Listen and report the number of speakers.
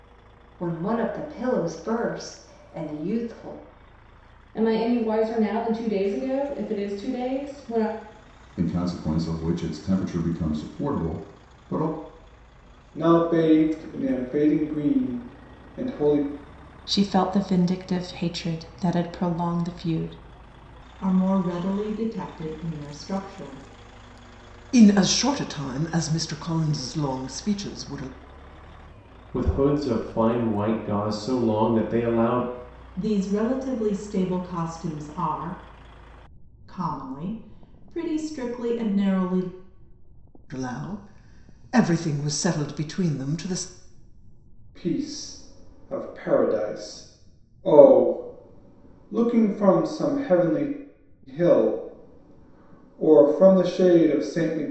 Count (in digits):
8